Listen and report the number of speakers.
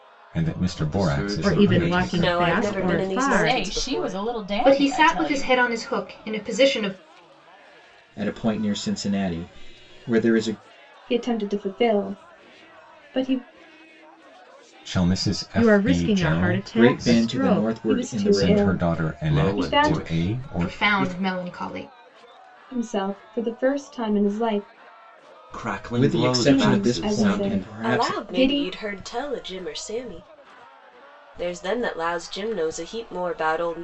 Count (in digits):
8